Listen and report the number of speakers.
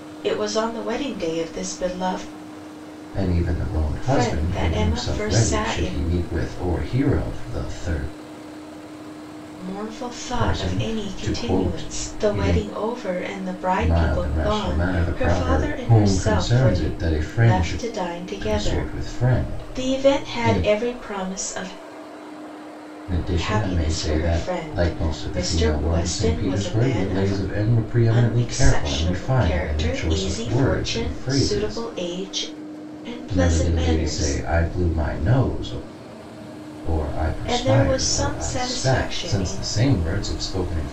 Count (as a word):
two